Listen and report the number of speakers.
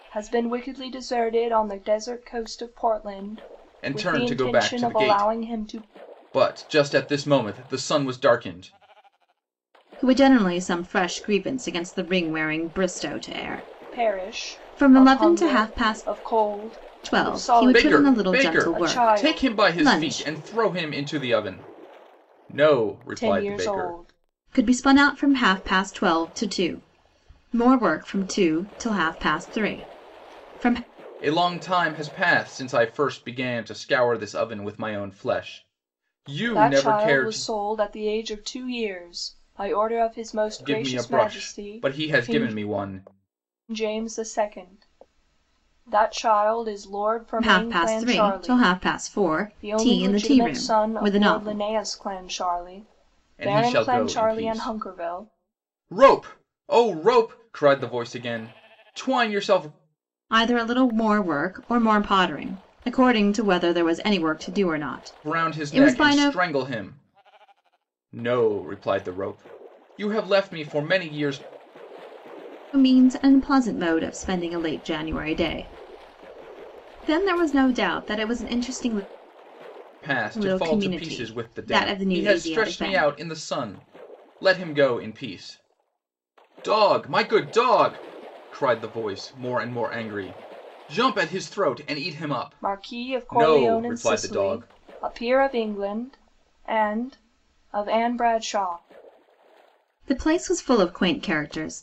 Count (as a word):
three